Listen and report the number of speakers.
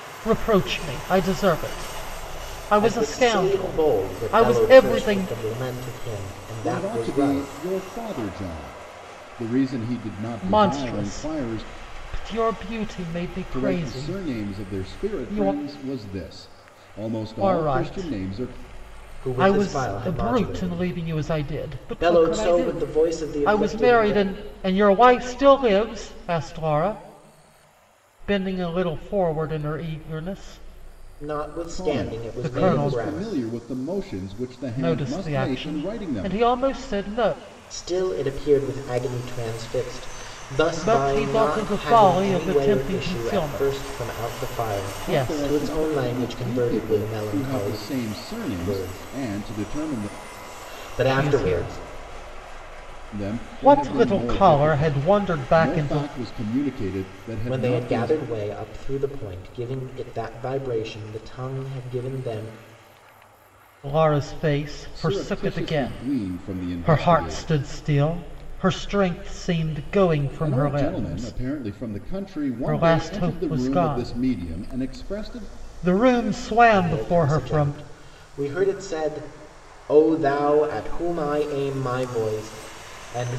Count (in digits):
3